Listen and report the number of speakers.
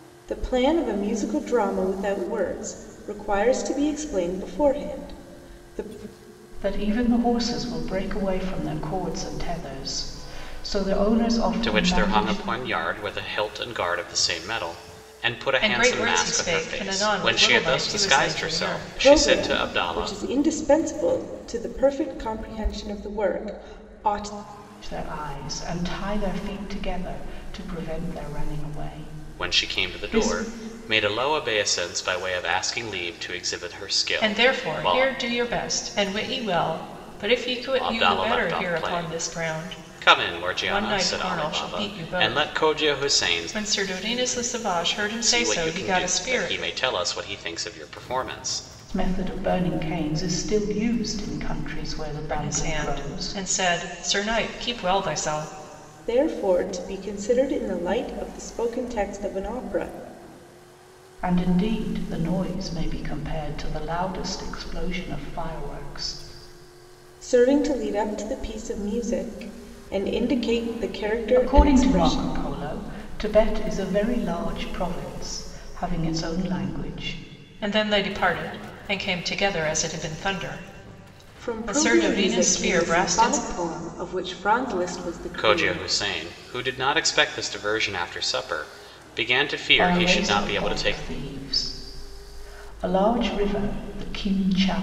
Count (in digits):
4